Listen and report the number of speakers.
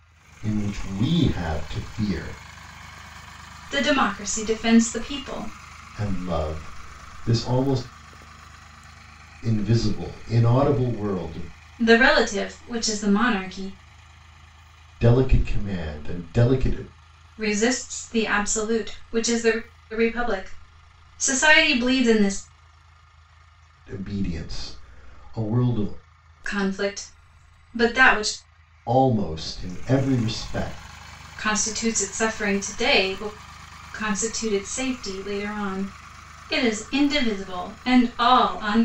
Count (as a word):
two